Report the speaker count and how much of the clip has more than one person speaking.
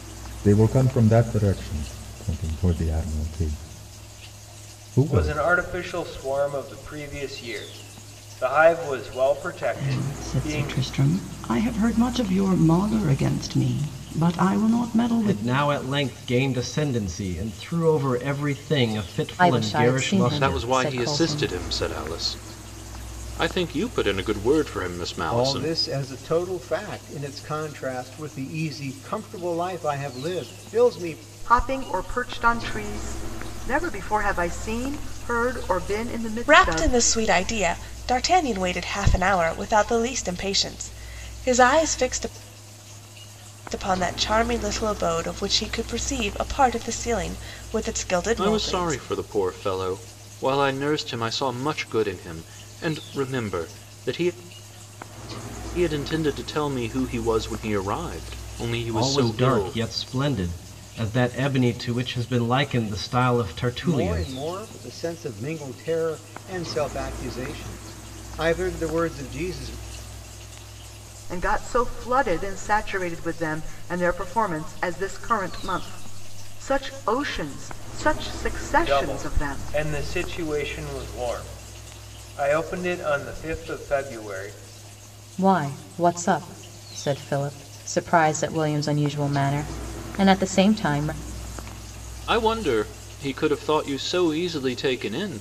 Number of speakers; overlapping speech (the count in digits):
9, about 8%